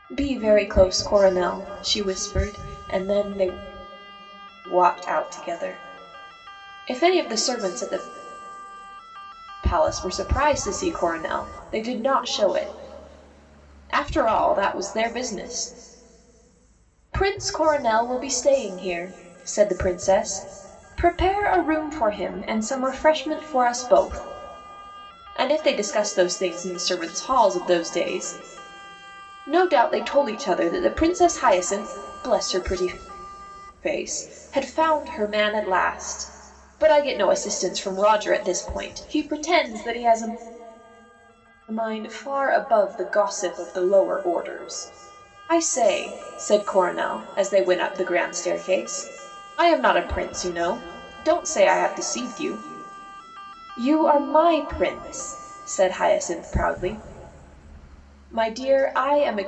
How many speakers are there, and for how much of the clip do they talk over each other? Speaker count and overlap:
one, no overlap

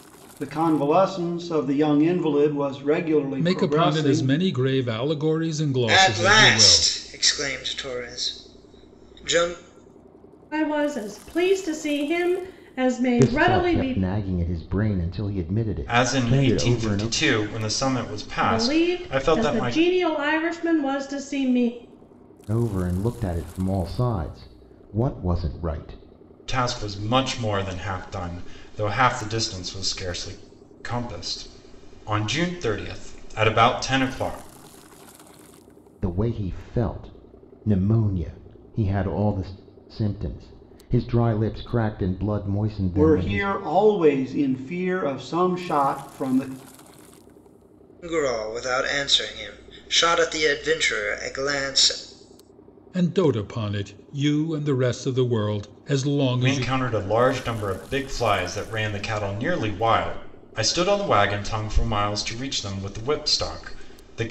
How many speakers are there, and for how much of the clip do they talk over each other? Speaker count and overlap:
six, about 10%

